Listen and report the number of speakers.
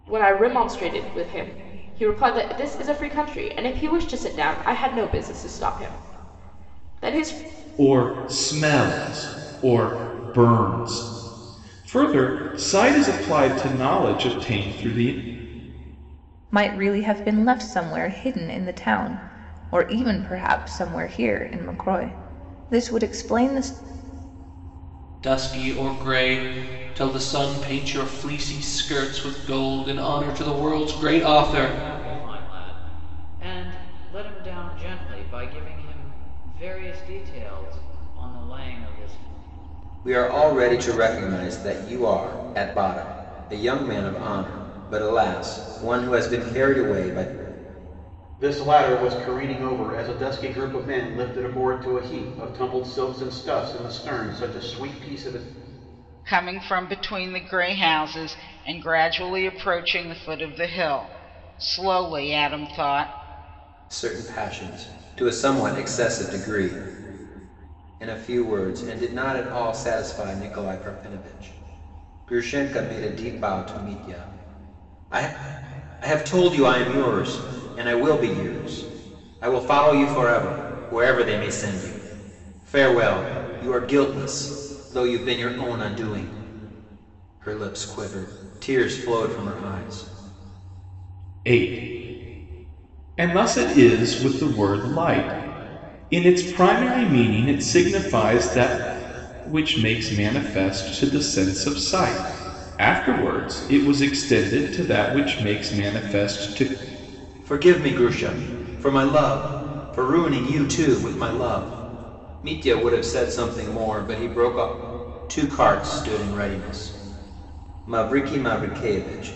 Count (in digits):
8